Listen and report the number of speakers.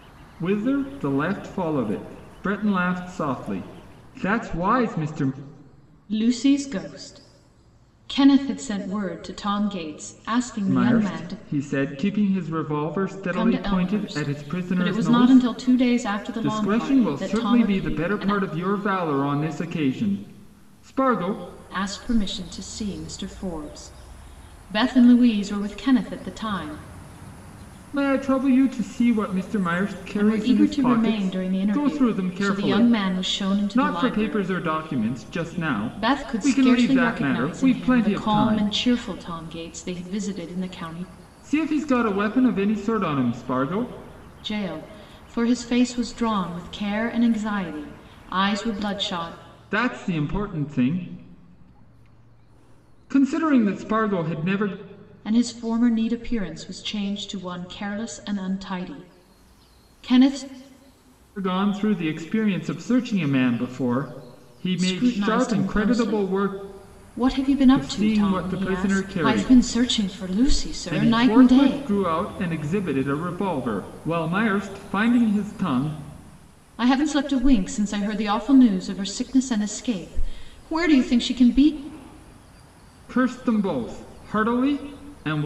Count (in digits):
2